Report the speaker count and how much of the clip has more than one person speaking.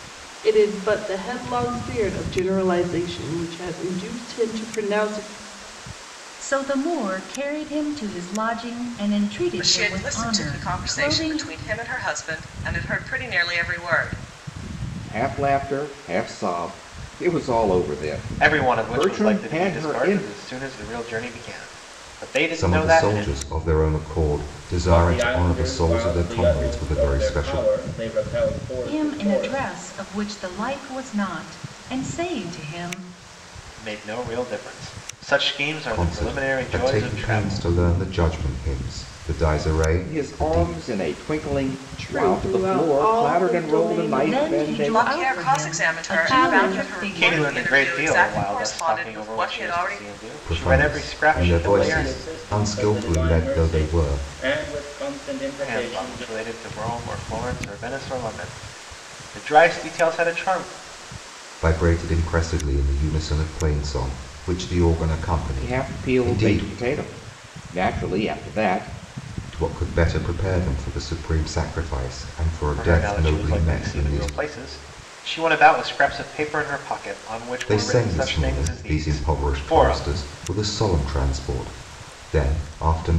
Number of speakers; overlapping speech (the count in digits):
7, about 35%